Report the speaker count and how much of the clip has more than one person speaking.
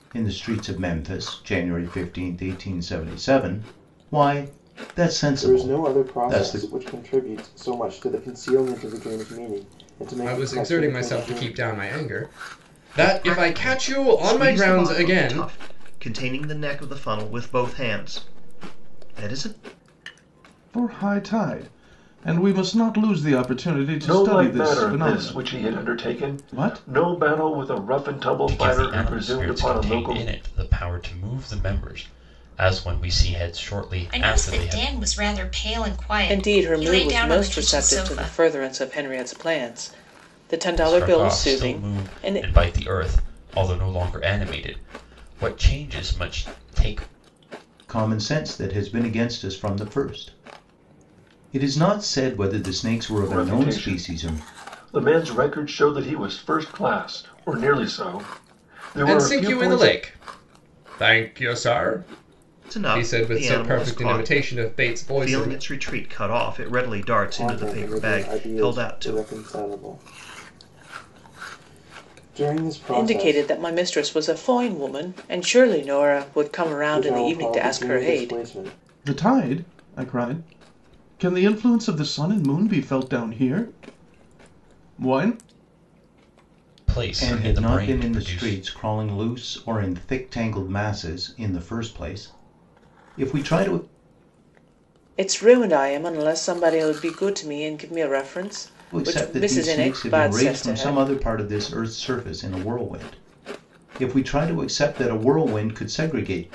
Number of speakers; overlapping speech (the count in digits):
9, about 25%